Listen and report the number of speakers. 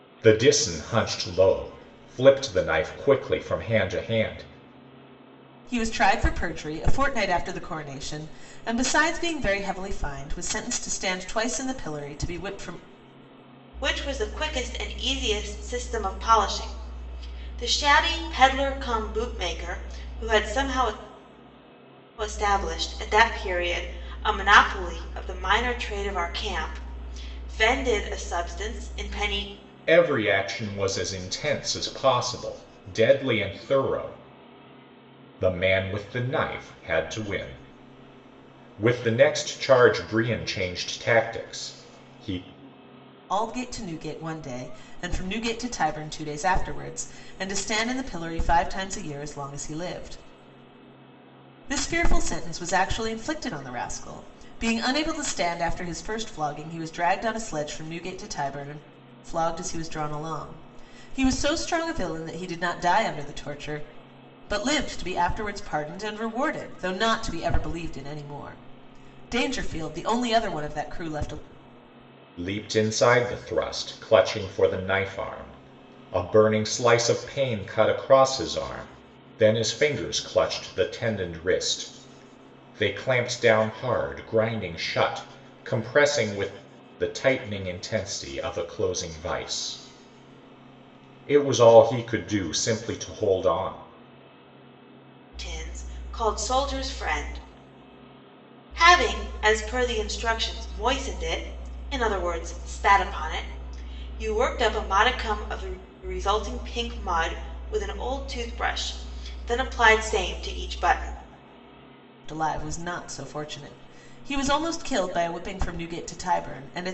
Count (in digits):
3